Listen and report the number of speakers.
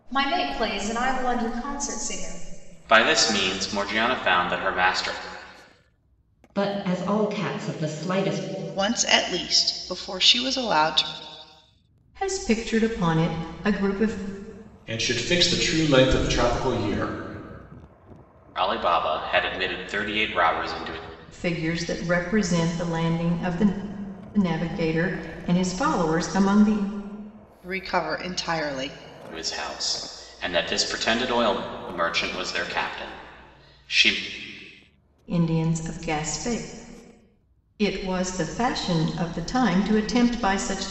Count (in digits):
6